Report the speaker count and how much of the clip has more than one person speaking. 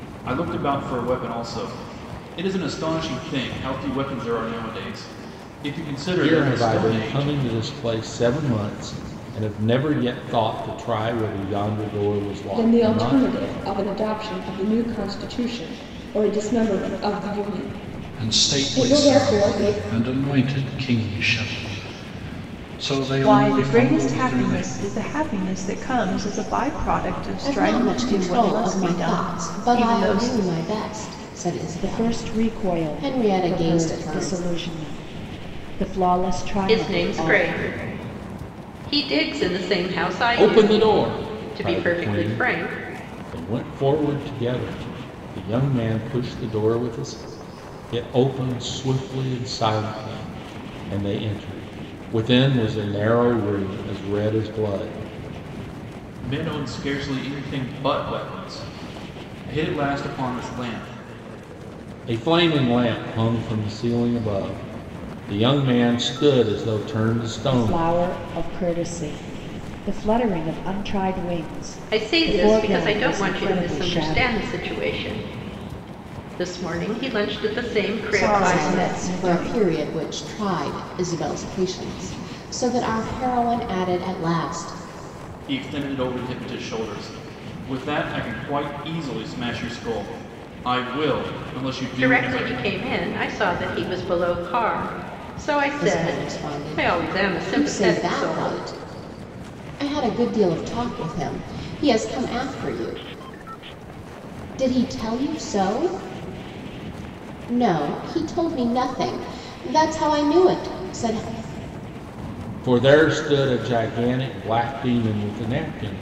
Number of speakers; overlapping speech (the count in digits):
8, about 19%